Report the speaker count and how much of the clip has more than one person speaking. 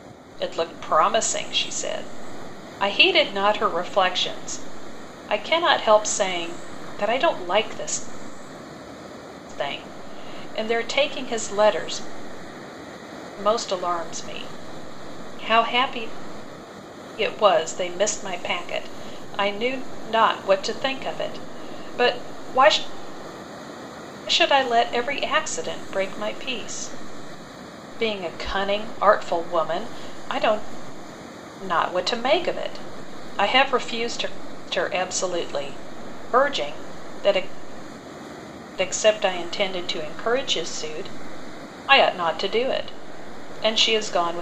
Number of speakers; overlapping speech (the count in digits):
1, no overlap